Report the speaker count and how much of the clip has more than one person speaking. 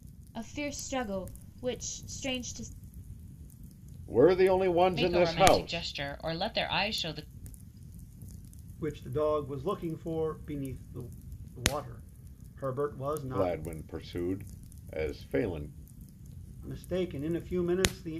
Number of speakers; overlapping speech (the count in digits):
4, about 7%